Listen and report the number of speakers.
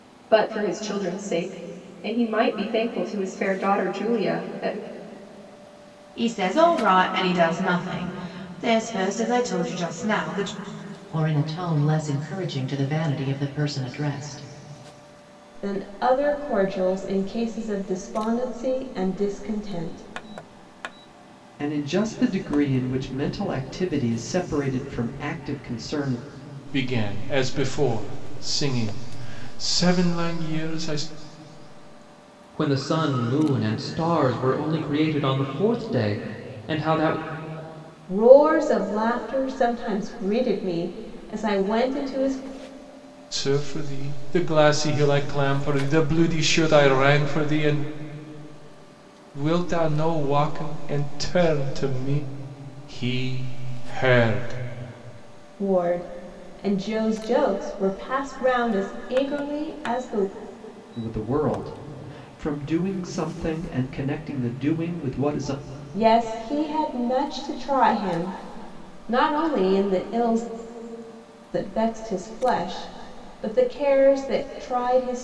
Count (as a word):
seven